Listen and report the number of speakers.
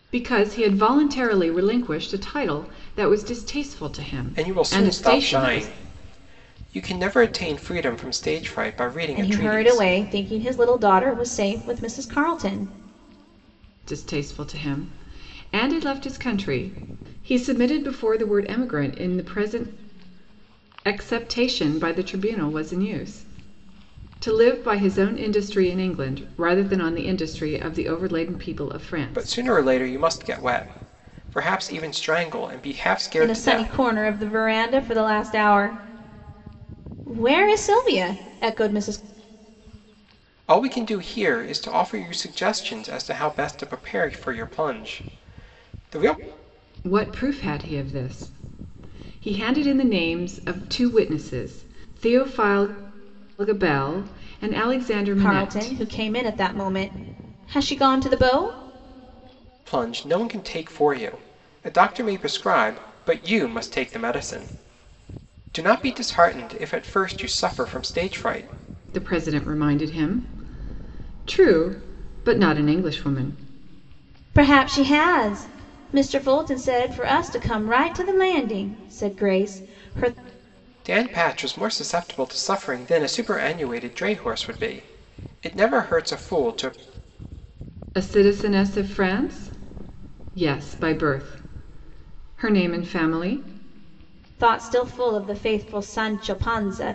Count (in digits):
3